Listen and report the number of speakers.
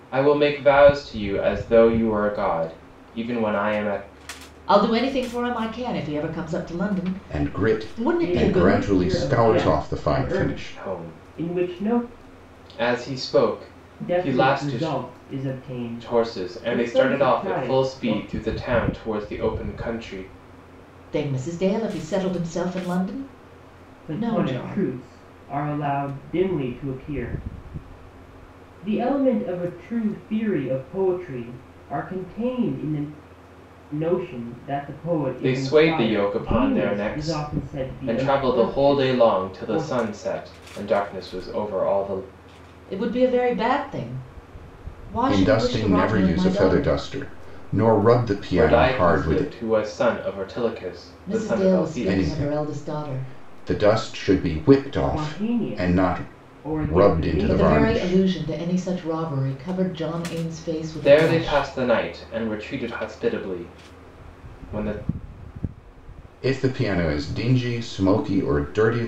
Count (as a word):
four